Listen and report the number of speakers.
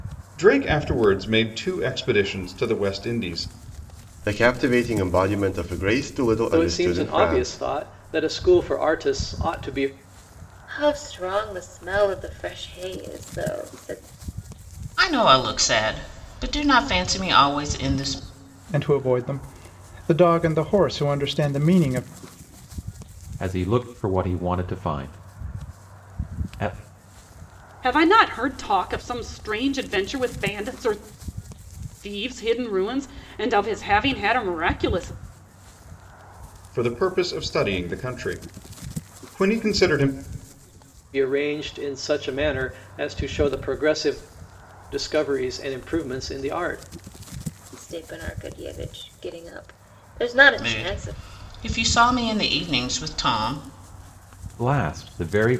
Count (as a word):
eight